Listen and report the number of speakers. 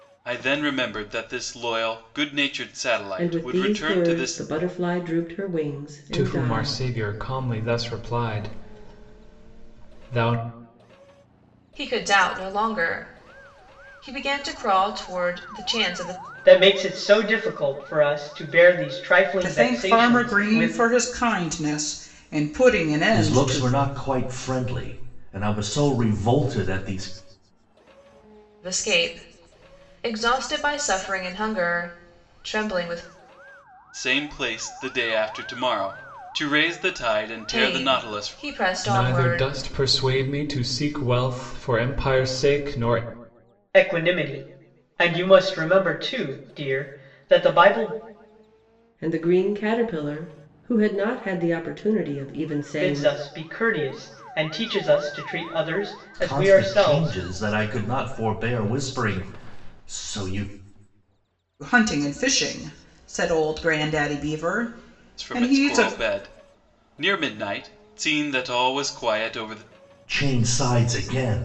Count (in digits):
7